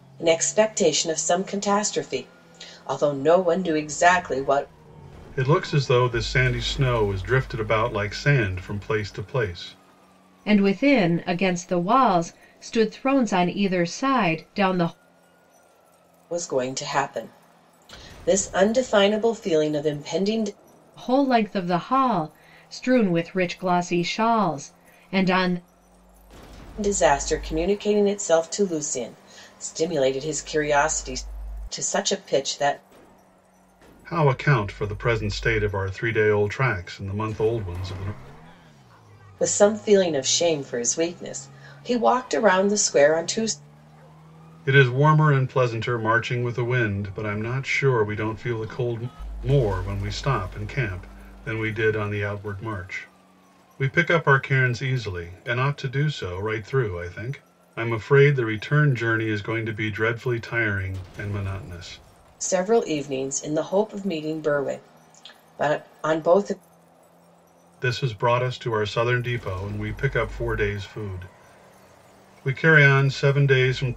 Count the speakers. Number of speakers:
three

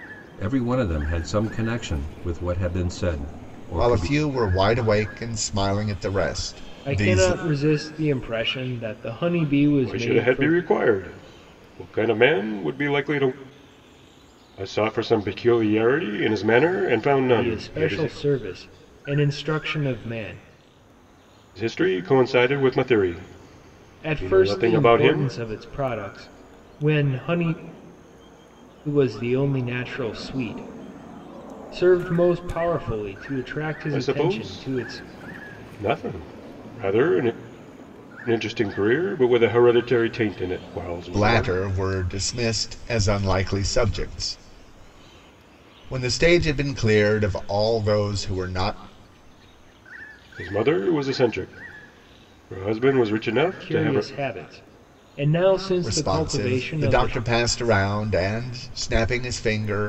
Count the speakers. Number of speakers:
four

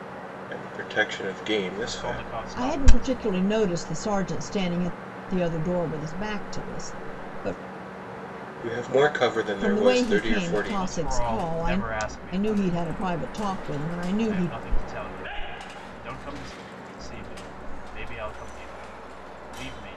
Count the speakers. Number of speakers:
three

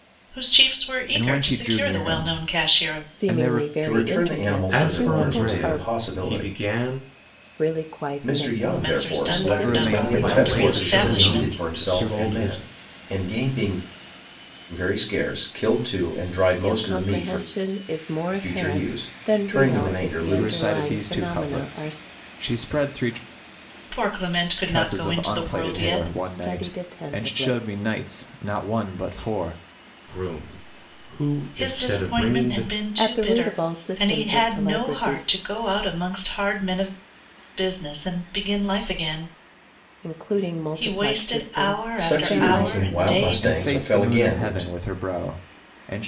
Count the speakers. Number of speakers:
five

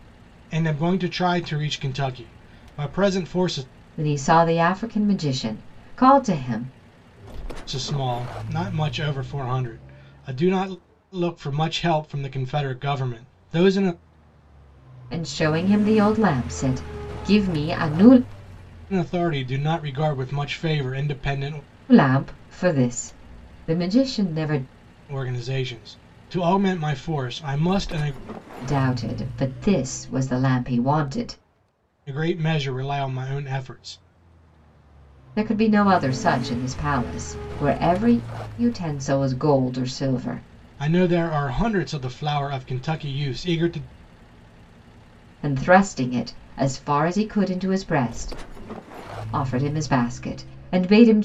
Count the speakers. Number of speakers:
two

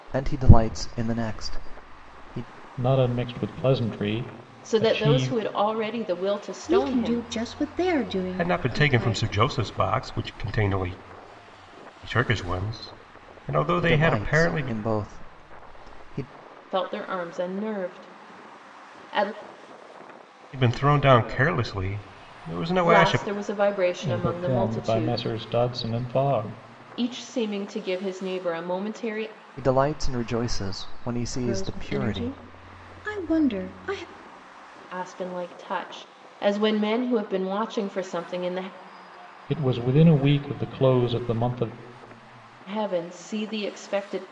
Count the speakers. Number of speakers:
five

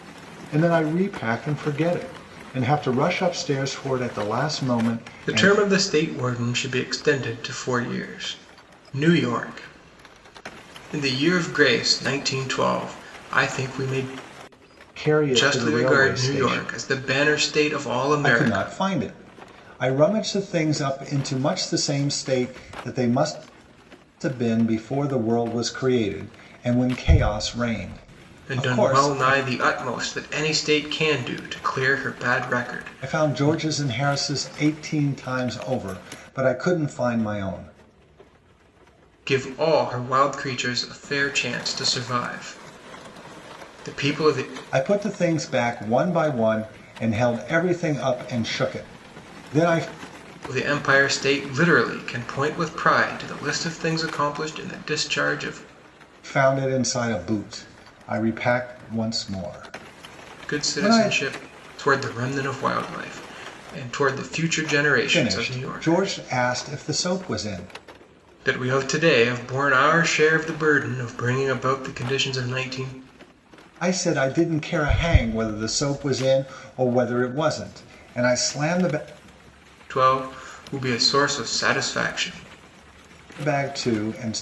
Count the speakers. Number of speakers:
two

